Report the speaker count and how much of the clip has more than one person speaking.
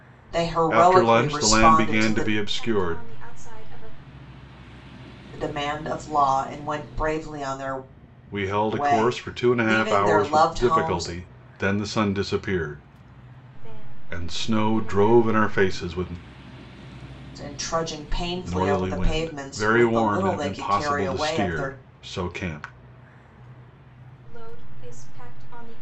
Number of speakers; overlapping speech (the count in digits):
3, about 38%